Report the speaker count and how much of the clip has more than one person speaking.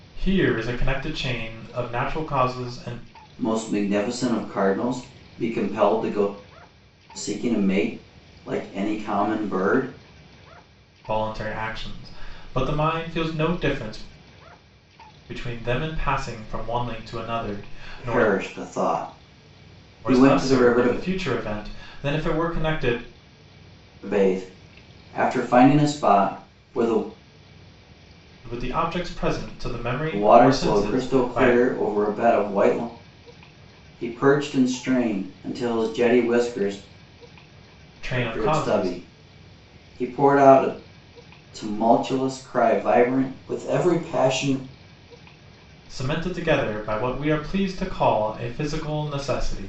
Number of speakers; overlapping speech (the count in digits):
2, about 7%